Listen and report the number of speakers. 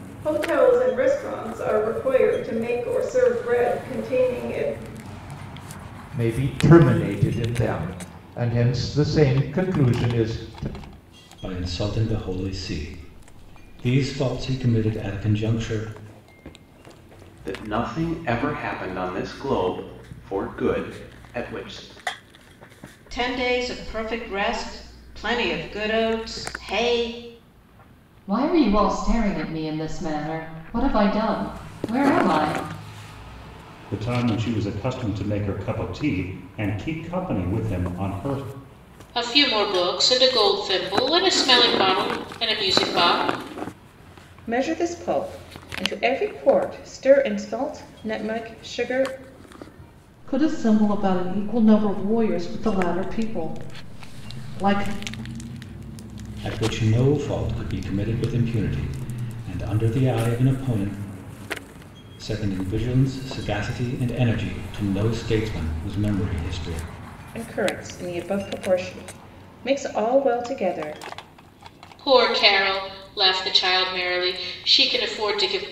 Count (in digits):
10